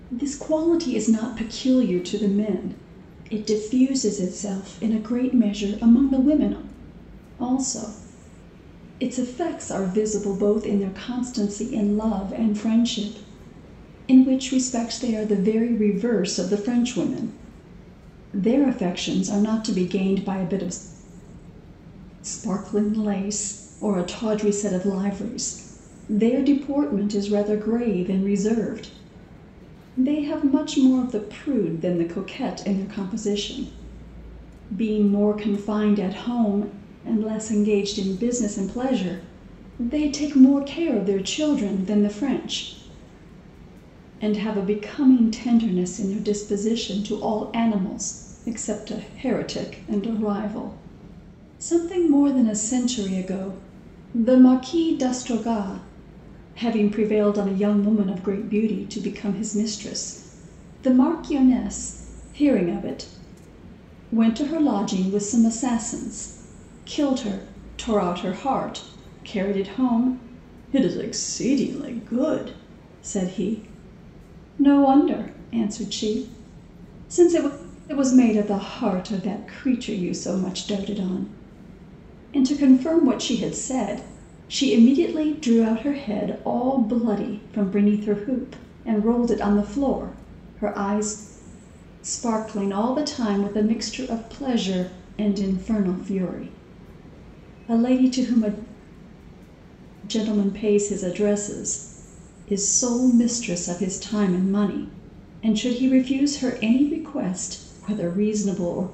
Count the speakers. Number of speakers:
one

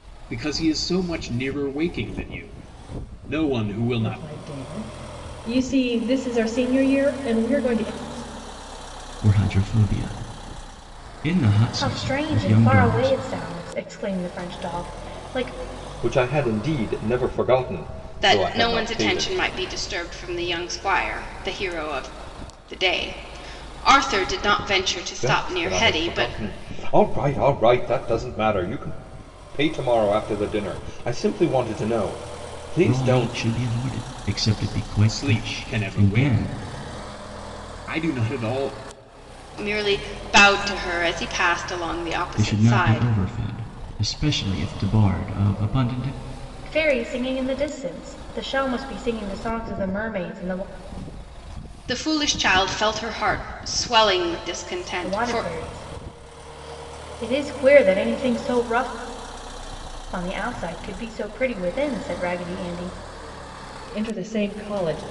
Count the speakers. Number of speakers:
six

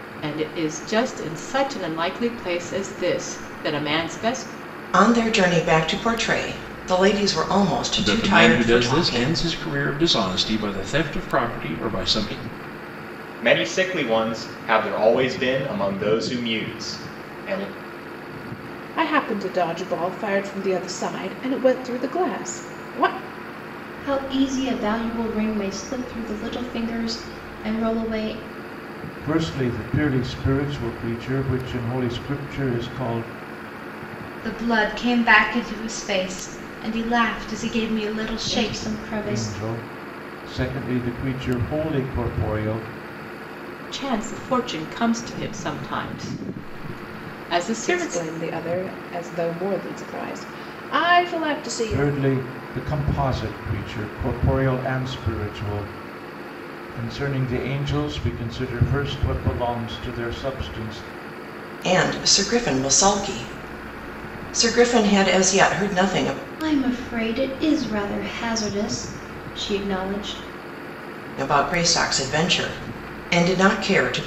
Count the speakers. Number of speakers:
eight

